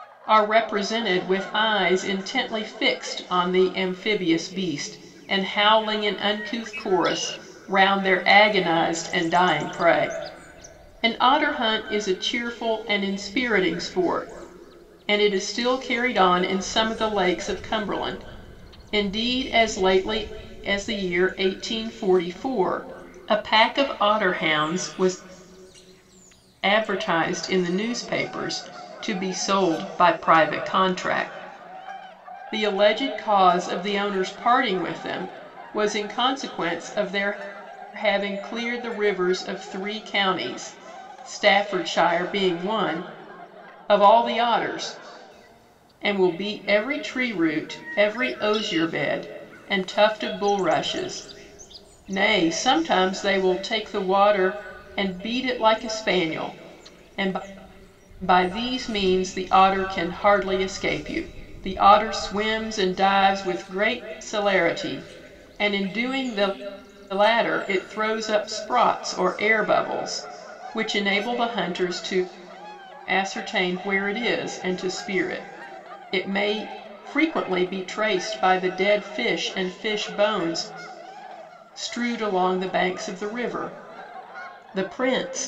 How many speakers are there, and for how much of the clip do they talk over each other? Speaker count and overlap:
one, no overlap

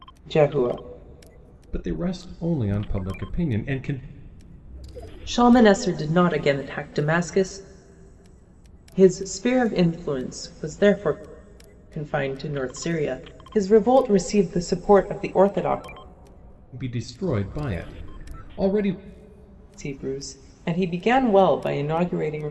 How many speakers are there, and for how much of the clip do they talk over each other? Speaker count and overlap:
two, no overlap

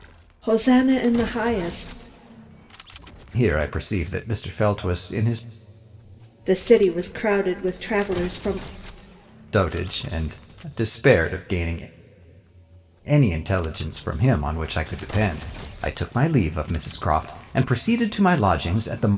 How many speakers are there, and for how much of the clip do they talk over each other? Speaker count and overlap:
two, no overlap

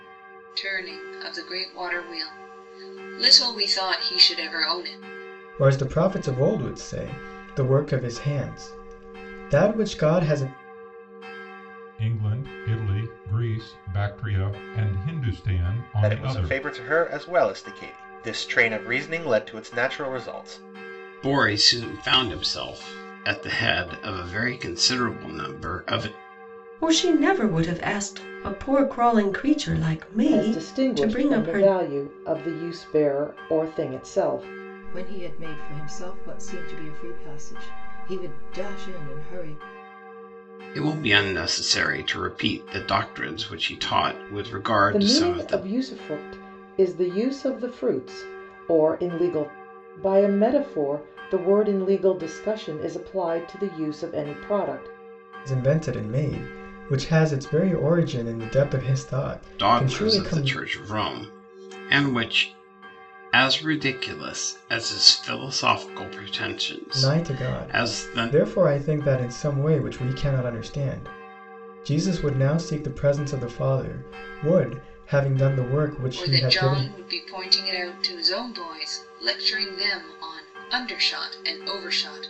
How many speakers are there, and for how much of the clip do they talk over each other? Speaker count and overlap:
eight, about 7%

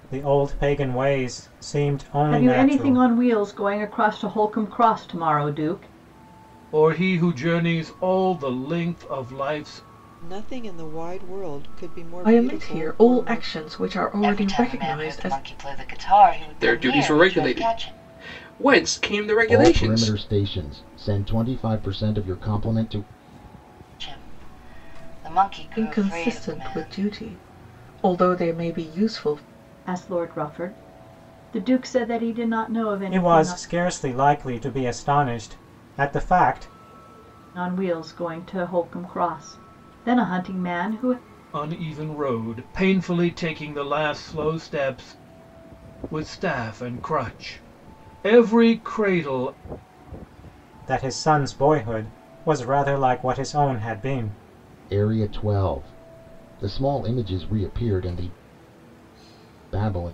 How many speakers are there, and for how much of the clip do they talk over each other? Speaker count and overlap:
eight, about 12%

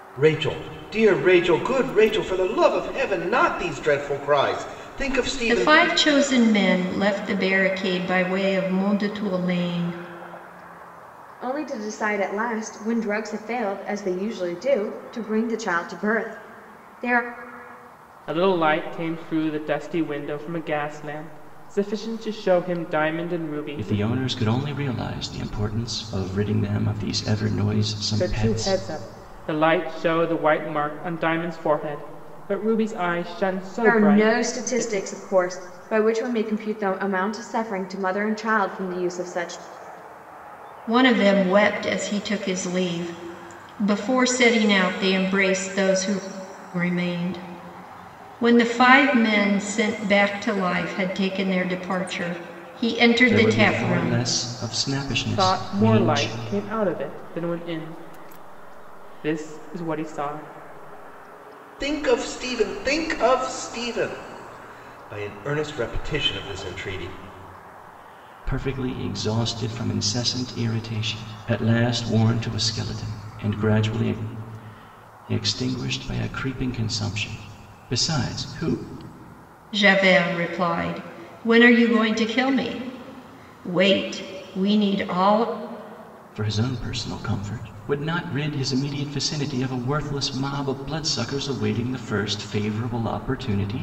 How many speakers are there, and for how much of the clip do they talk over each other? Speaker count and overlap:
five, about 5%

